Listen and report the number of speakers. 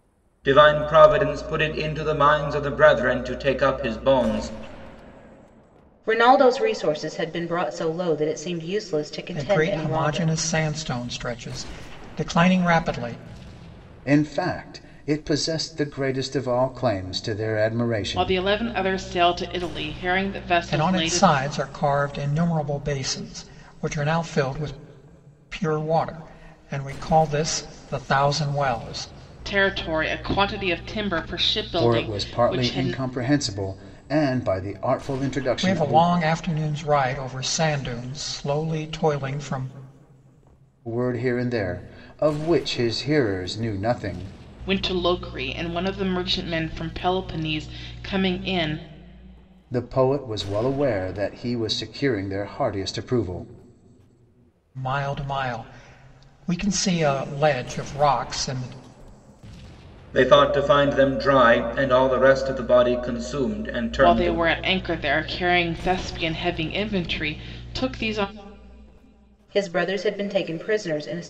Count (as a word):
five